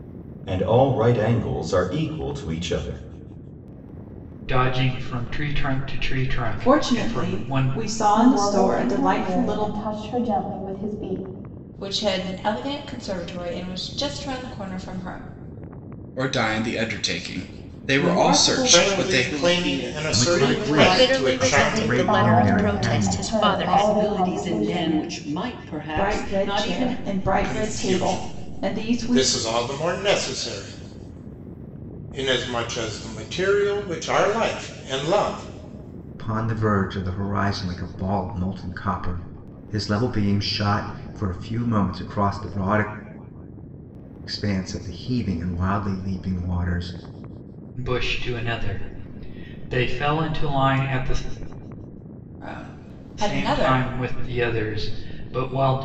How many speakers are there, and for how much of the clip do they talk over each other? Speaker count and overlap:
10, about 25%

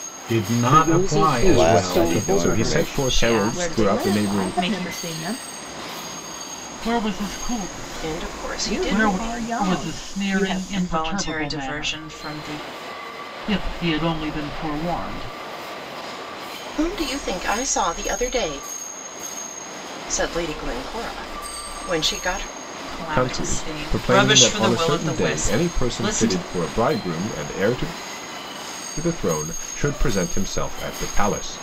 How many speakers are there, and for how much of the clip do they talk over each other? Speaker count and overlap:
8, about 37%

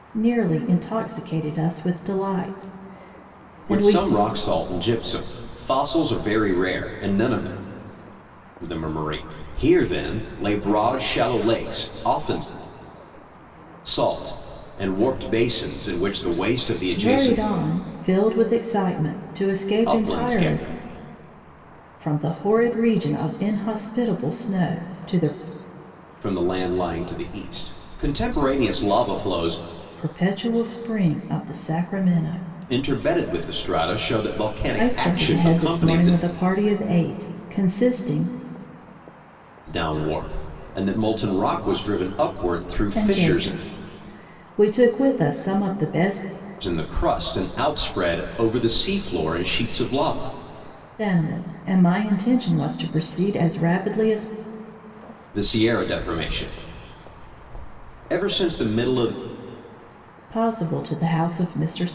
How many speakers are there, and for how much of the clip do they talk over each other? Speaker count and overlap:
2, about 6%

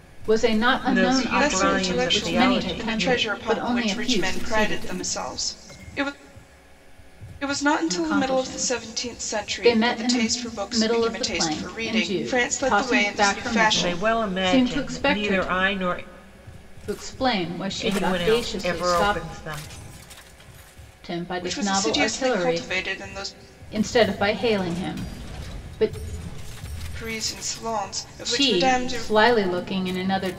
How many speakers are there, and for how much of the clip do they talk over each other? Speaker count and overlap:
3, about 50%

